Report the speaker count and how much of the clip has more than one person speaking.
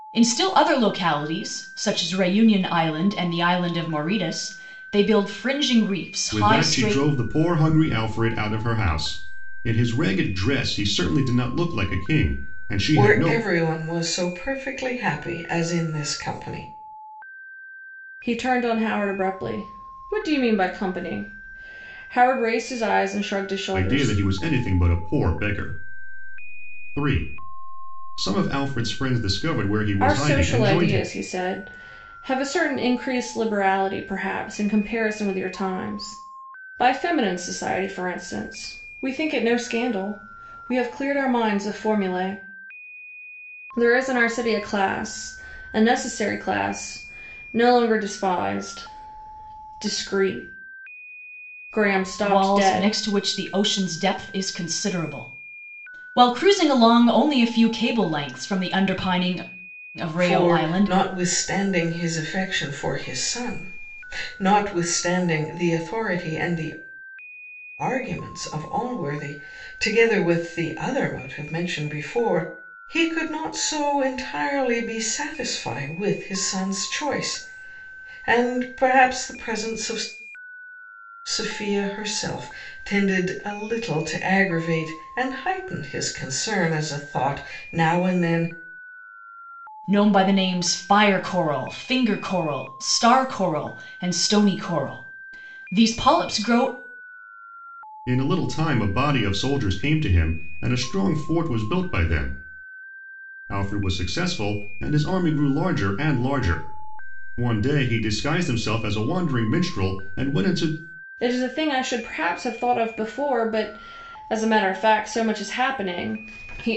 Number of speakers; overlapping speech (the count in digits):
4, about 4%